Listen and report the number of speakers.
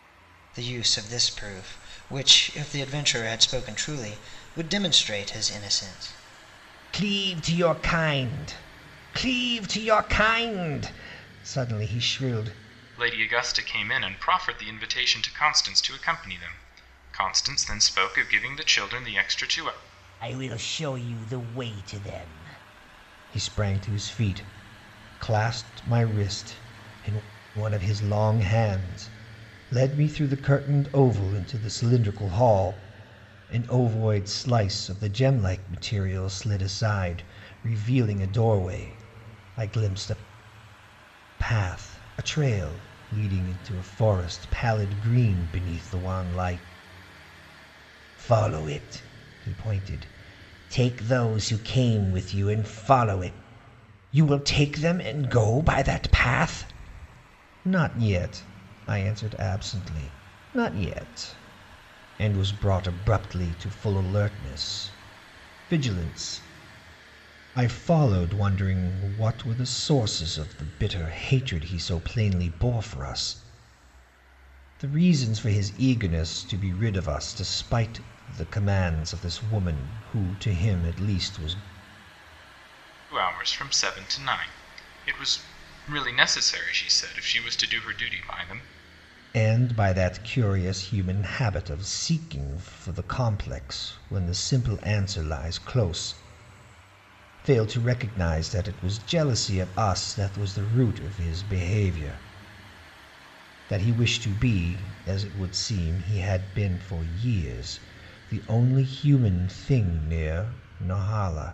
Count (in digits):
3